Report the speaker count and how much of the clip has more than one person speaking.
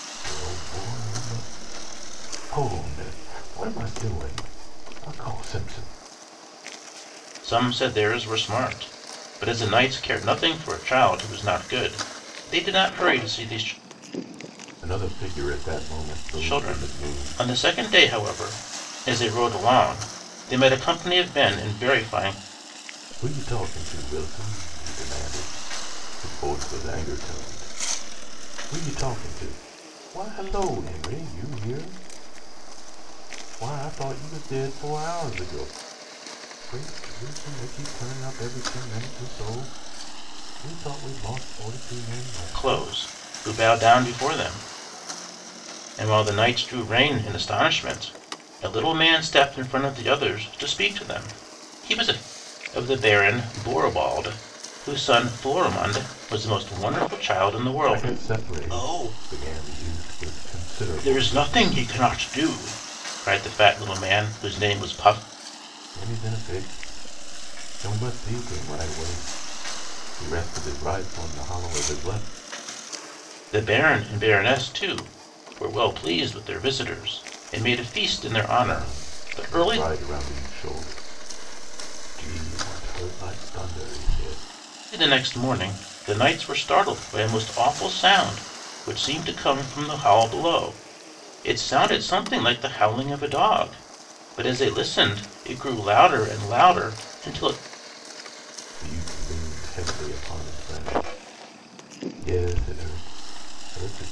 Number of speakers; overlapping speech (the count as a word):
two, about 5%